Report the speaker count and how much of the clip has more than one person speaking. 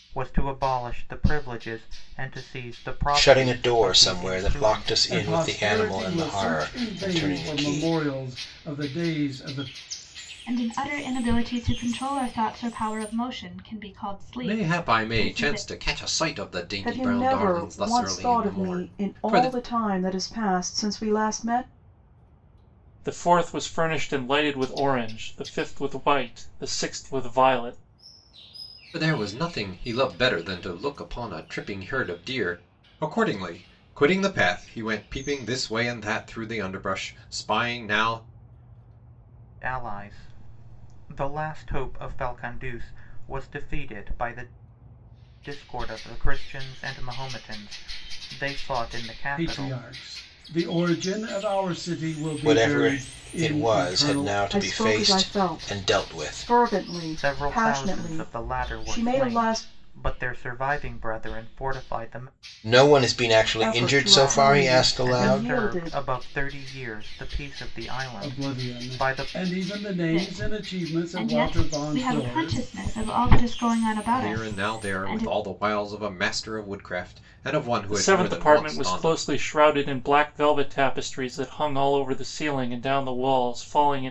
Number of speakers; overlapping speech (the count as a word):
seven, about 29%